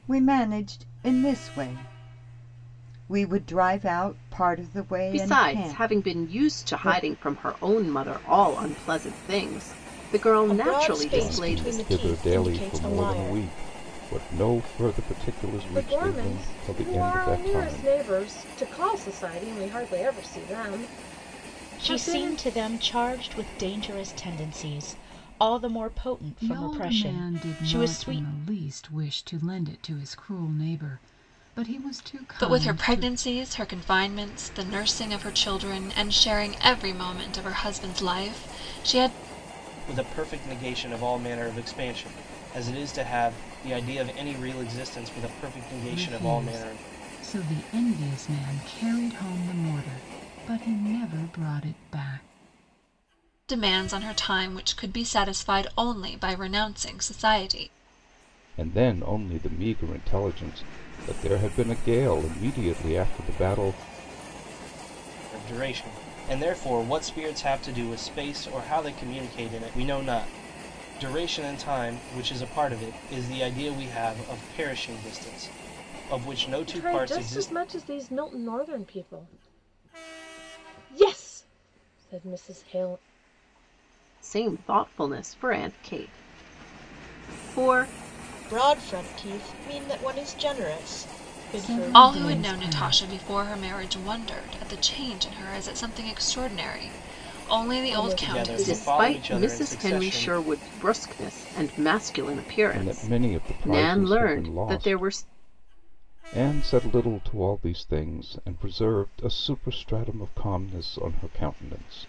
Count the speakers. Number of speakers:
nine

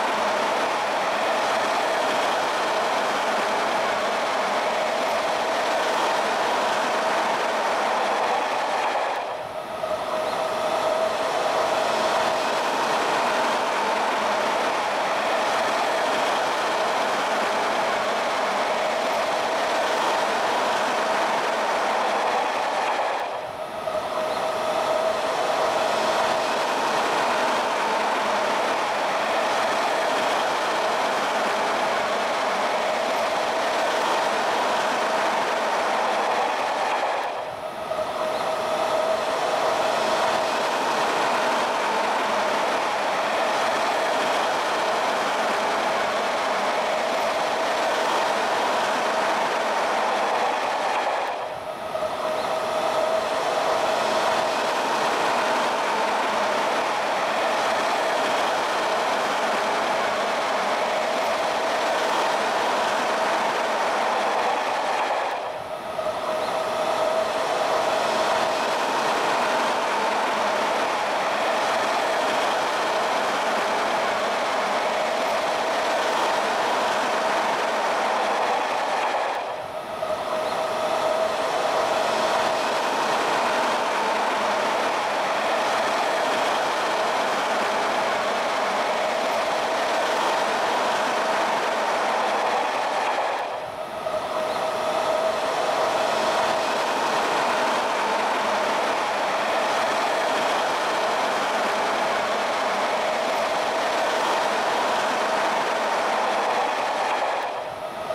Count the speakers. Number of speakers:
zero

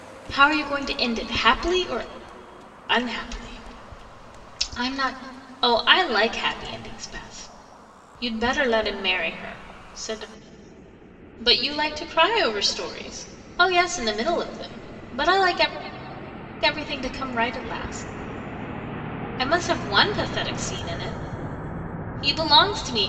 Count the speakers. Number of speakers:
one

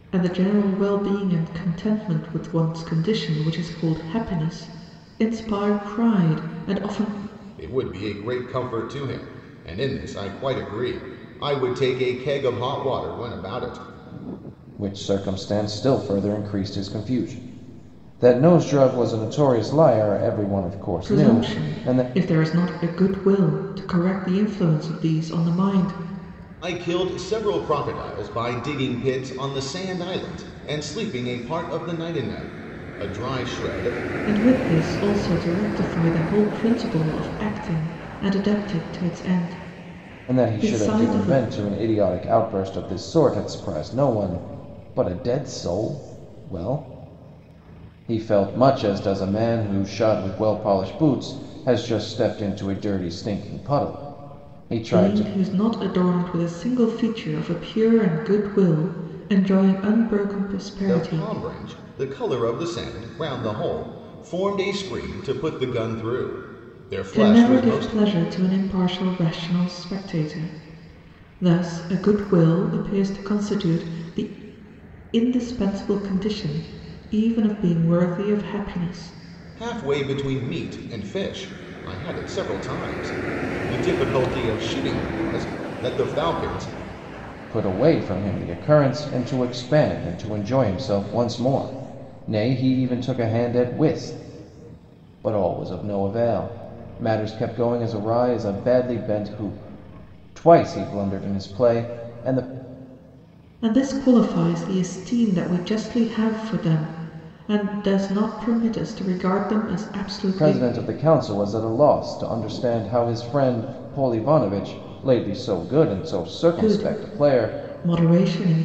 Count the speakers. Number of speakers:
three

